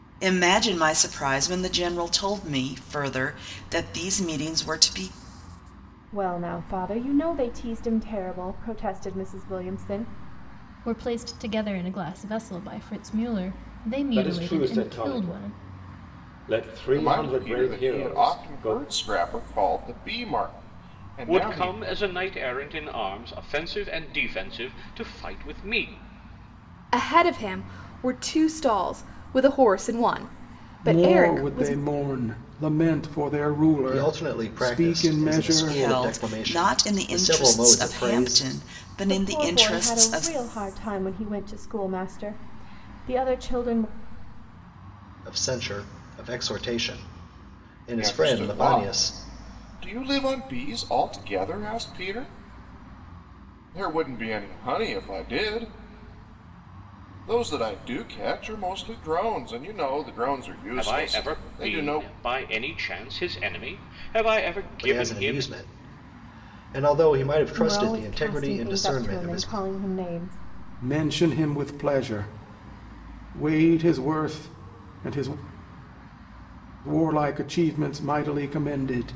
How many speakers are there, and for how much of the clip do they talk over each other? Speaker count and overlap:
9, about 20%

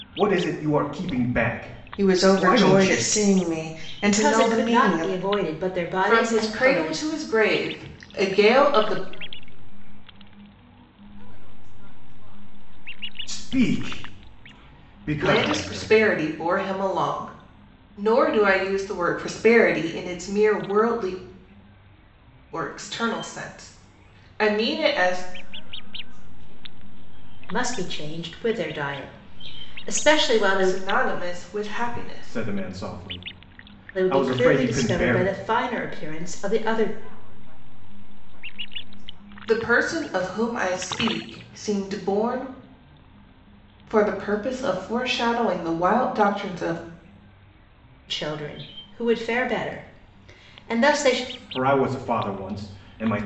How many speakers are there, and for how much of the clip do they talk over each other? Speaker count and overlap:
5, about 23%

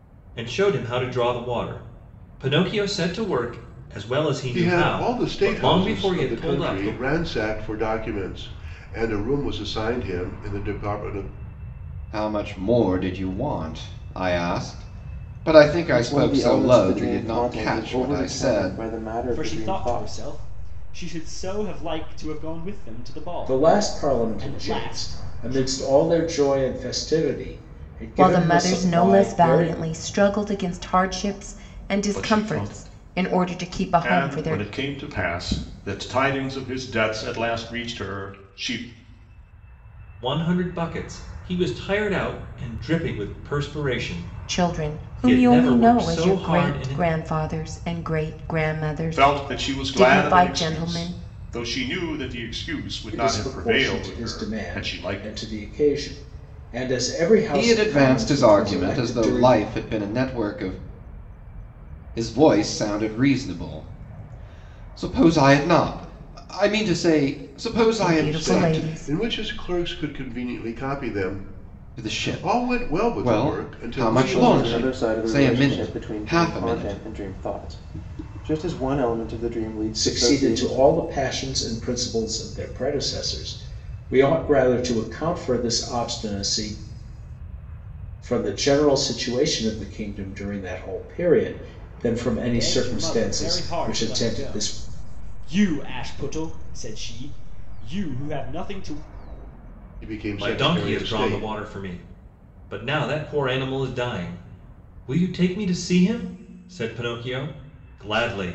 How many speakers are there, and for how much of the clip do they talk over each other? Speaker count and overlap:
8, about 30%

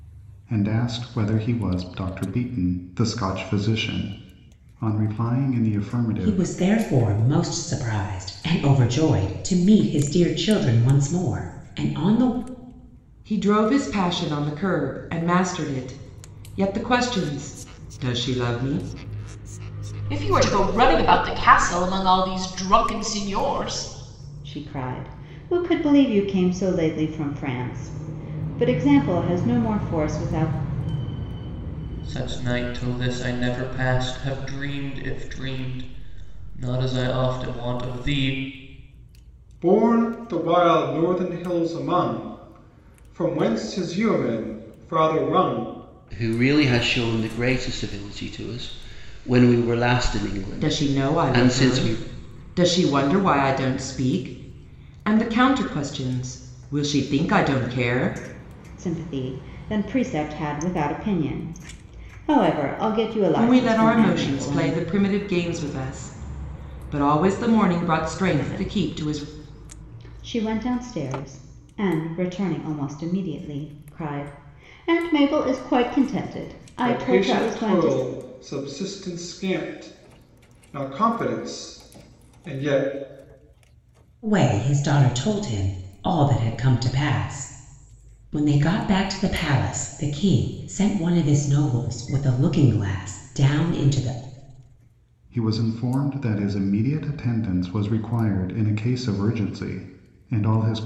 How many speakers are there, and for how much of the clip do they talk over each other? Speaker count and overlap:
8, about 5%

